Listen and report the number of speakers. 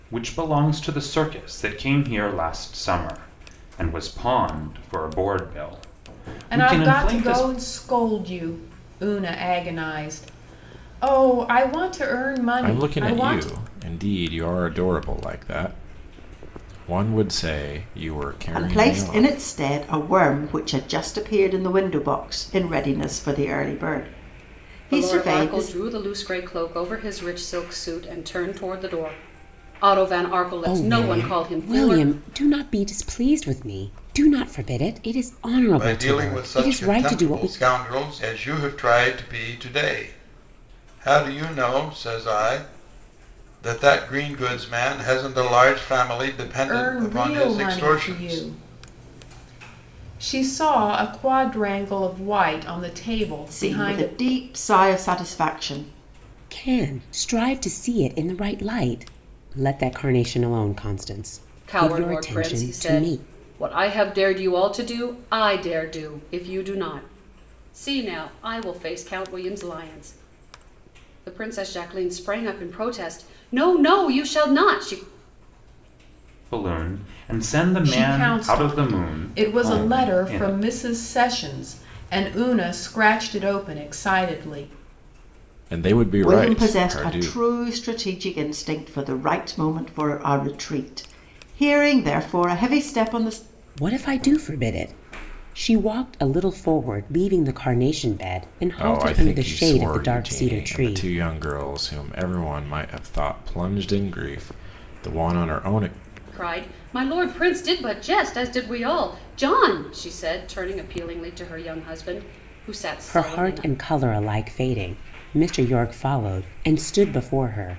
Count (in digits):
7